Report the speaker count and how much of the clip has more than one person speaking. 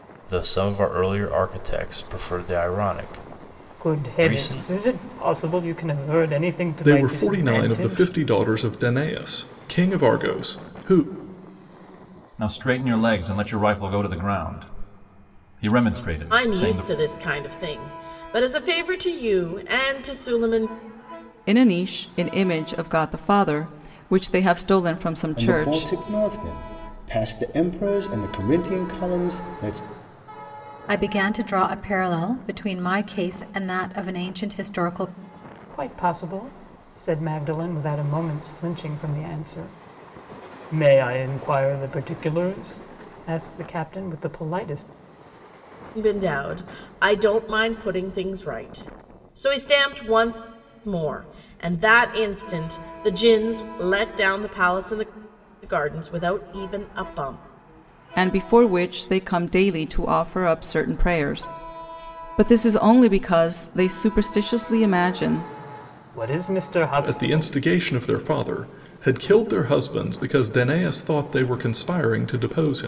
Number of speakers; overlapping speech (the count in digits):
8, about 6%